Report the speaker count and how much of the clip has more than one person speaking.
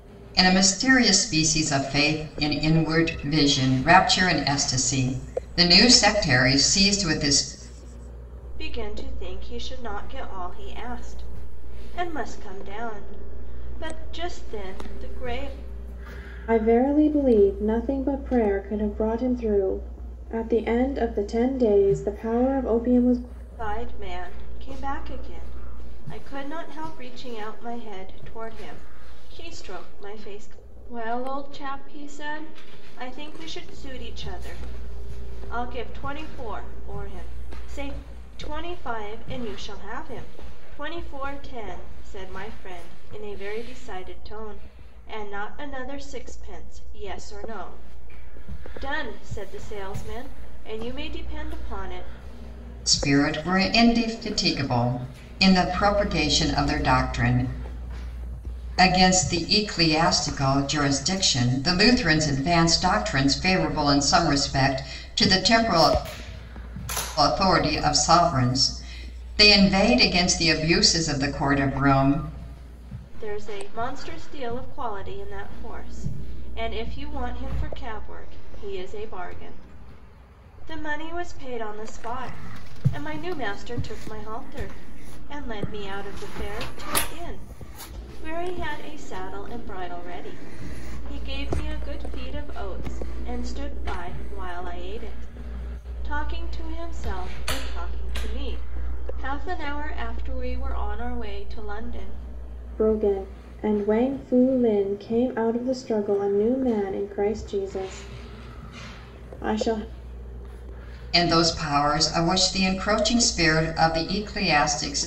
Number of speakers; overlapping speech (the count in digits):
3, no overlap